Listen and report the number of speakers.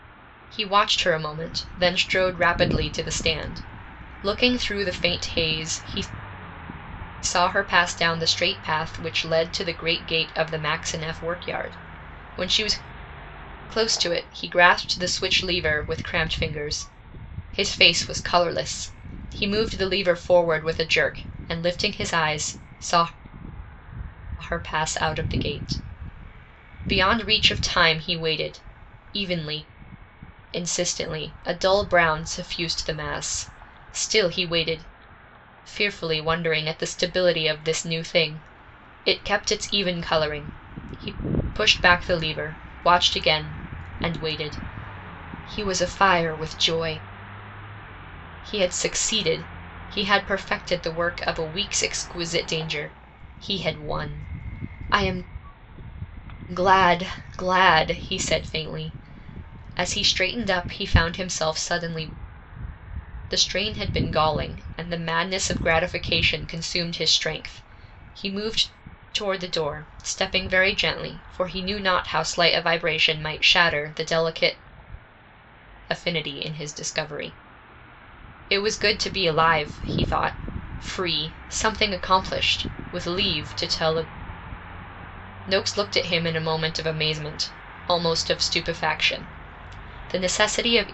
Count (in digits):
1